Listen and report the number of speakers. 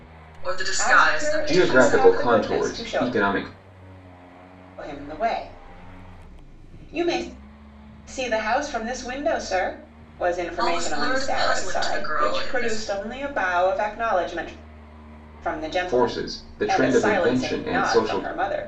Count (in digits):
3